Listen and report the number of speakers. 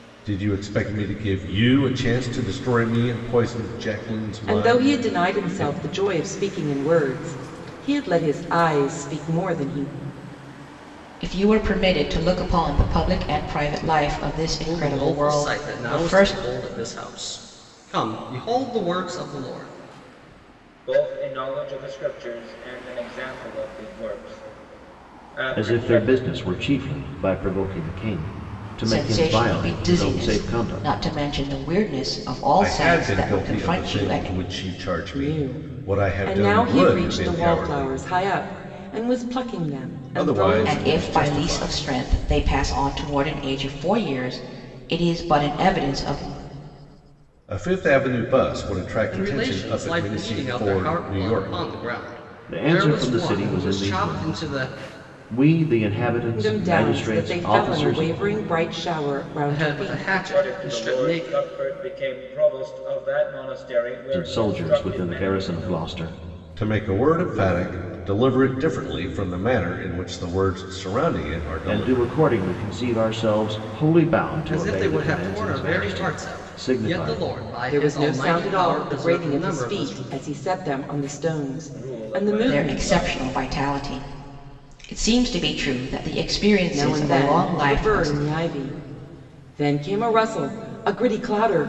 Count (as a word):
six